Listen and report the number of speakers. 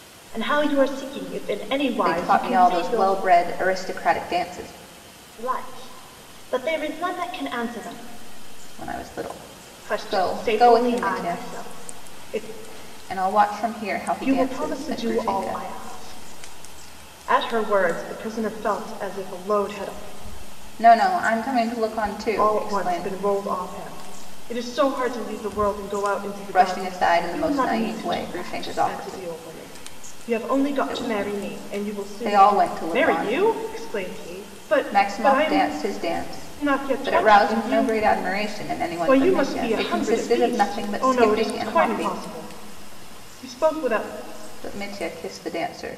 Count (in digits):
2